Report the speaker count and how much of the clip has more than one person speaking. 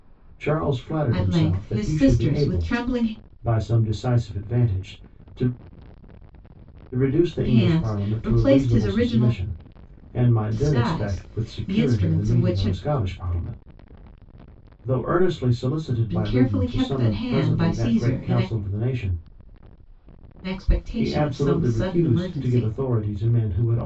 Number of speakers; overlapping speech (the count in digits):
2, about 43%